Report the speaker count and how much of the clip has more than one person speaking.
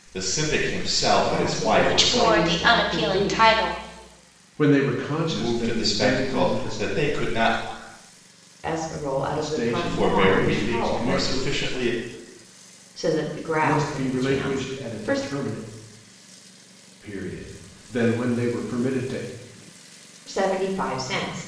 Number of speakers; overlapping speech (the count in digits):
4, about 36%